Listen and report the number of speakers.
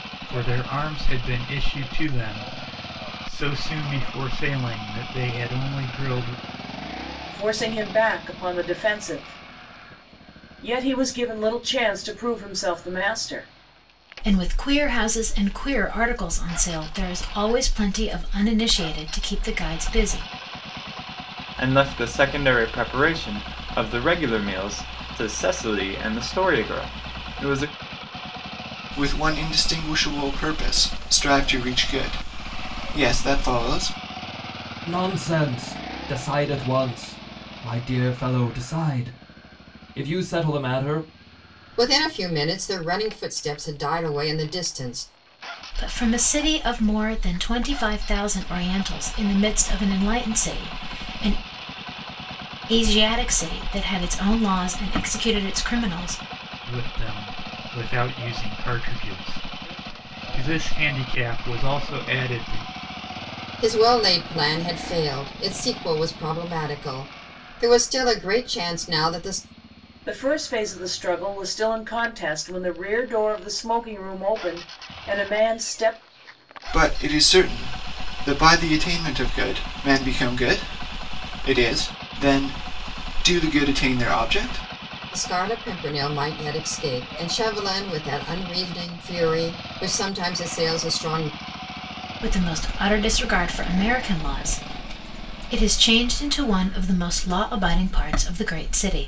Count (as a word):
seven